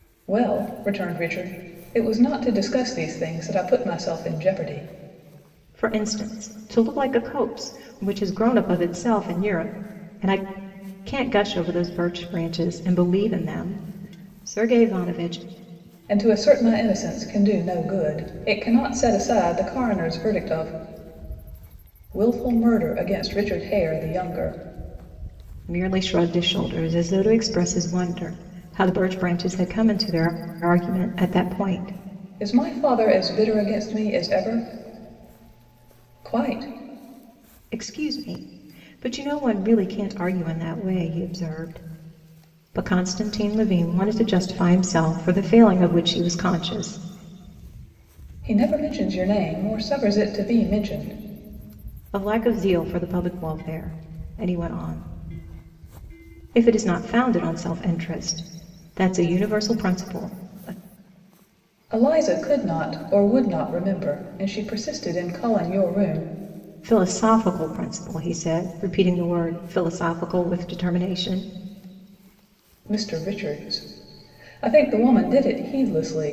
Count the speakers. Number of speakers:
two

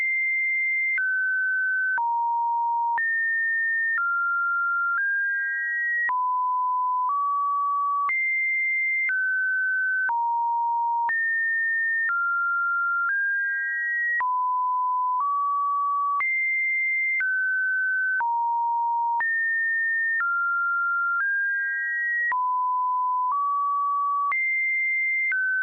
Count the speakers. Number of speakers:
zero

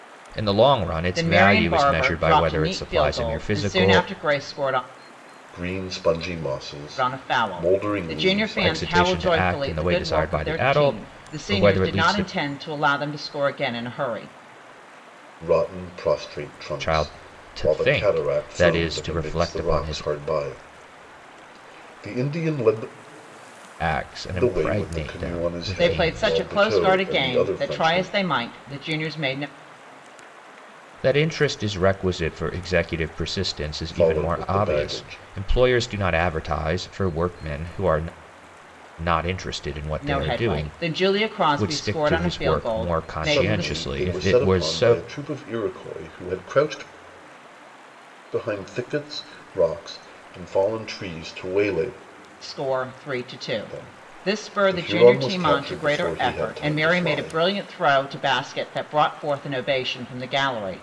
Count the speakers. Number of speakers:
three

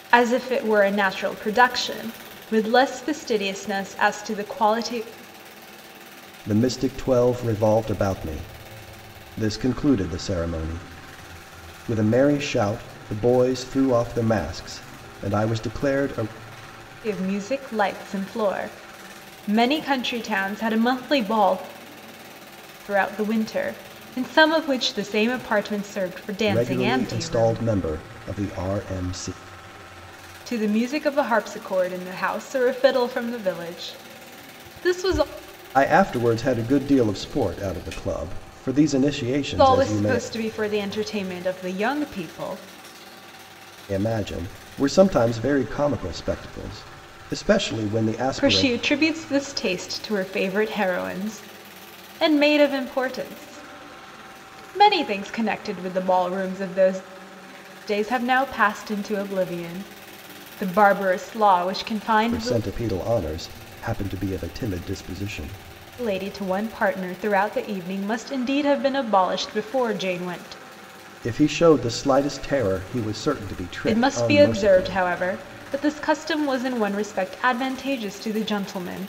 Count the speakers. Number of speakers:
two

